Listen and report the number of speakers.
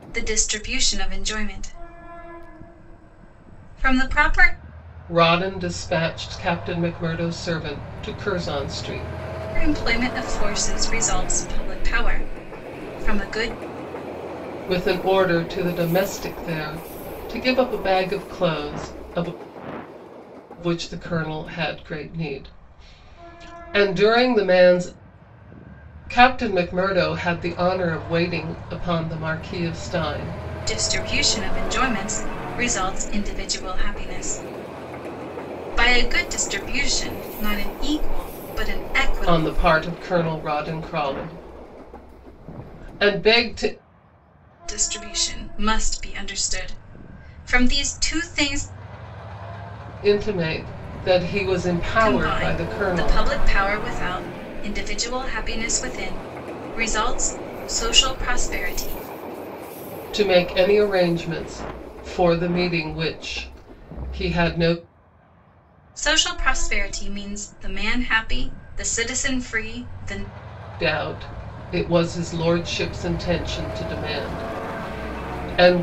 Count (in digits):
2